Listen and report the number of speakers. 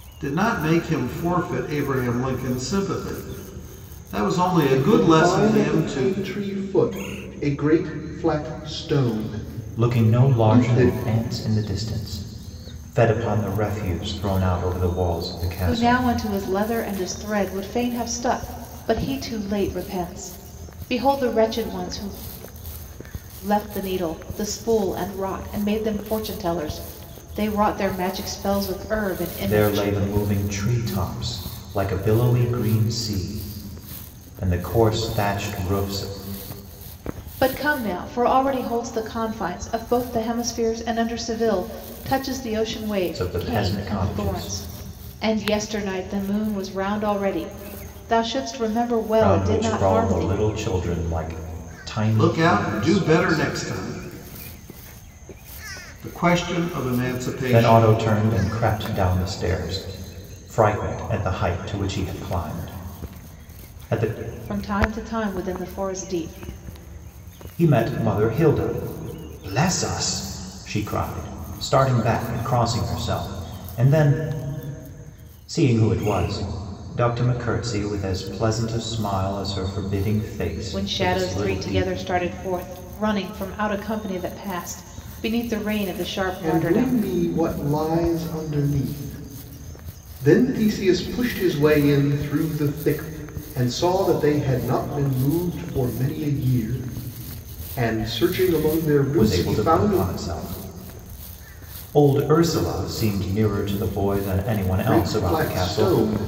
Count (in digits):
4